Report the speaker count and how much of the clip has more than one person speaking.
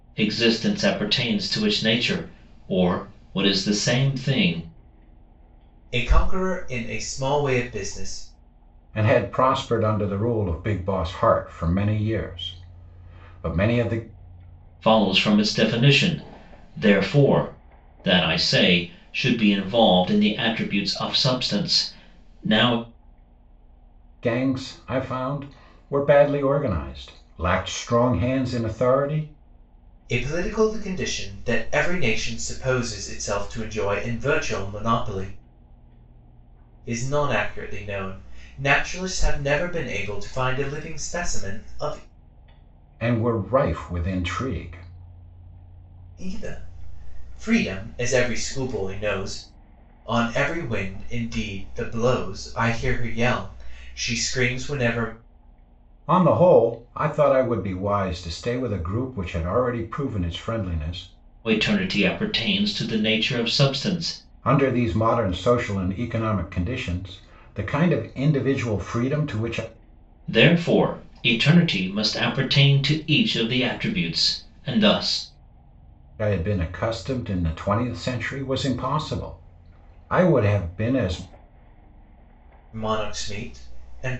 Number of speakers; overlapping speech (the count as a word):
three, no overlap